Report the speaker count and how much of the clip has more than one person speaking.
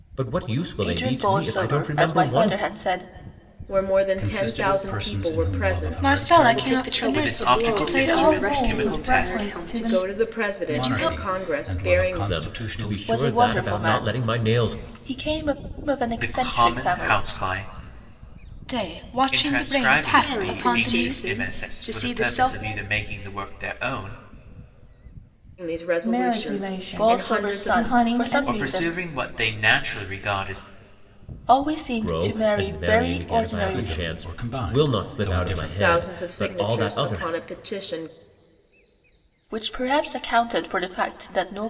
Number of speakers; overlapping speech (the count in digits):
8, about 60%